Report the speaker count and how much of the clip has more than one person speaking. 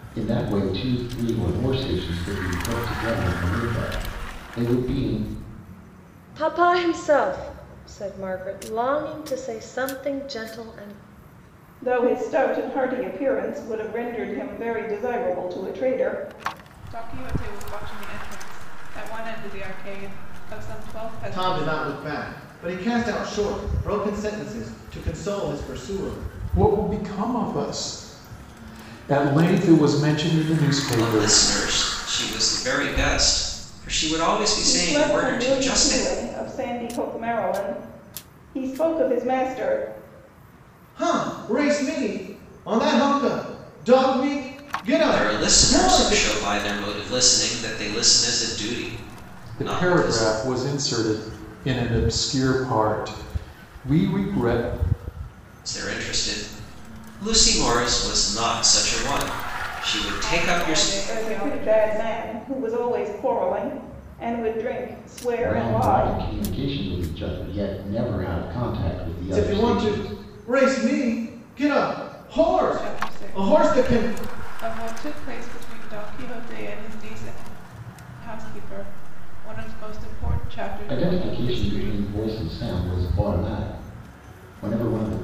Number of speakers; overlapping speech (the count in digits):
7, about 12%